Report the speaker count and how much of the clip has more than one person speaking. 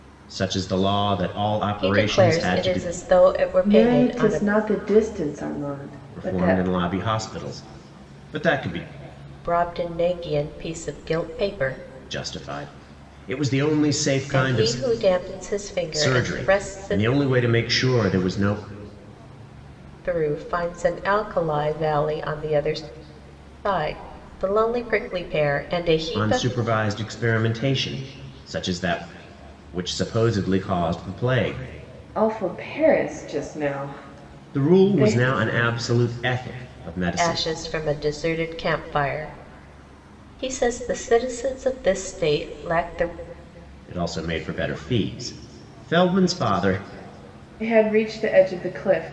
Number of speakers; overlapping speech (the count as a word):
three, about 12%